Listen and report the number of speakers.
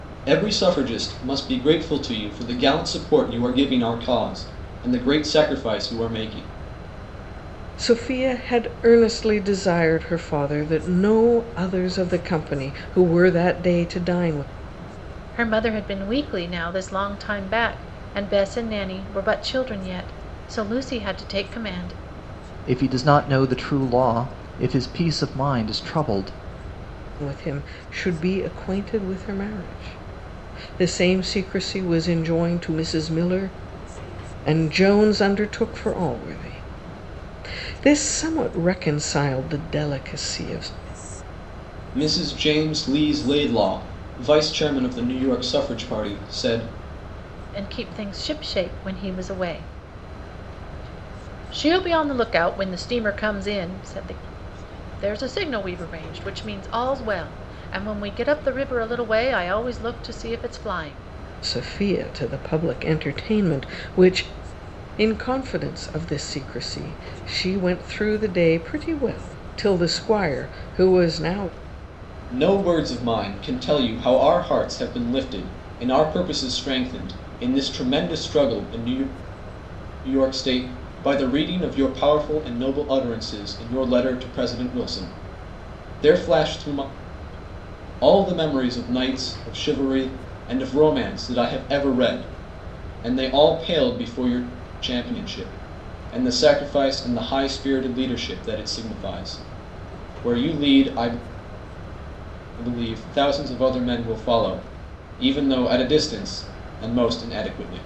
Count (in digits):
4